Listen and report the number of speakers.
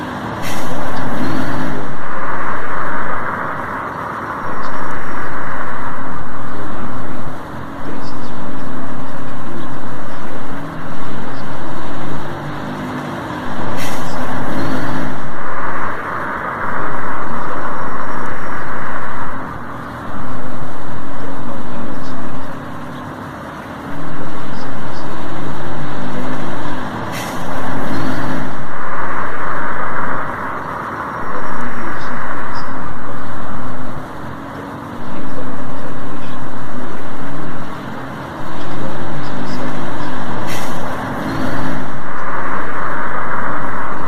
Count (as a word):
one